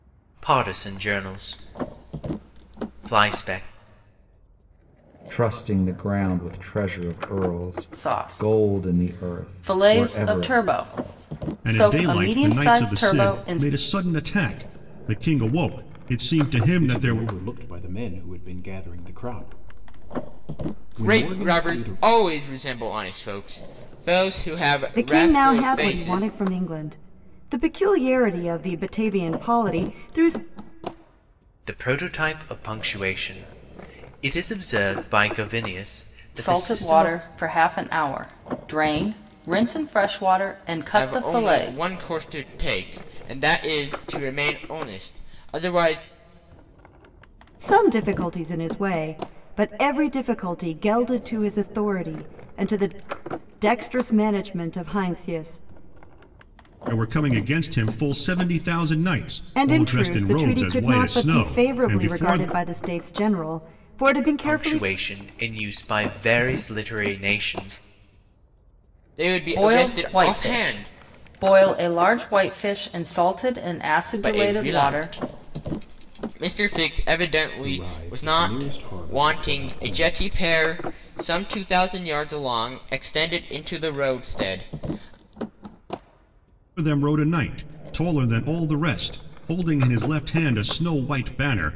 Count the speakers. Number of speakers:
7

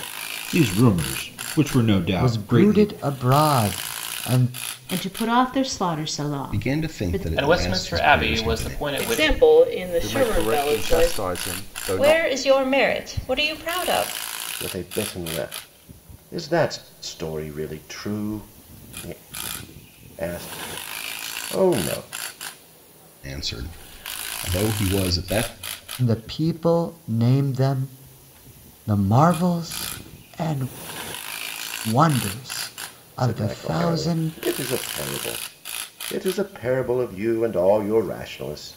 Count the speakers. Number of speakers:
9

